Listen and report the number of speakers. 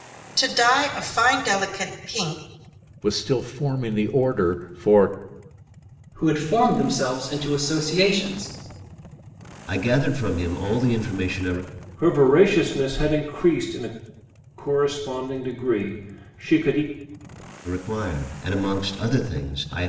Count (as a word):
five